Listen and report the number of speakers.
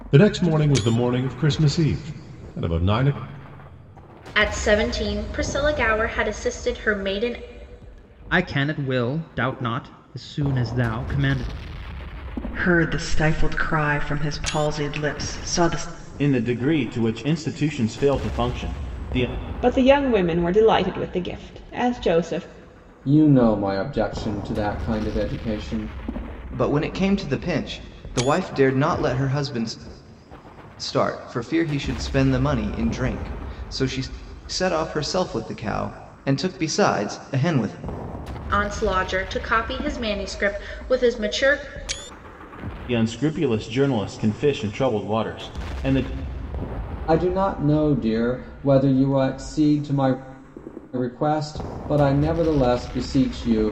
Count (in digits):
8